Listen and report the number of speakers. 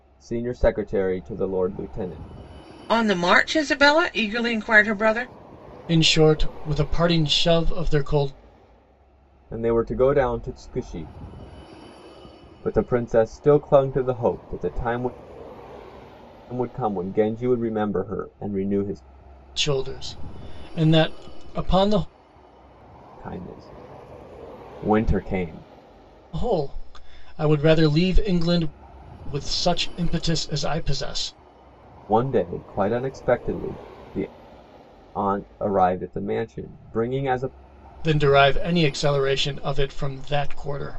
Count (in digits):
3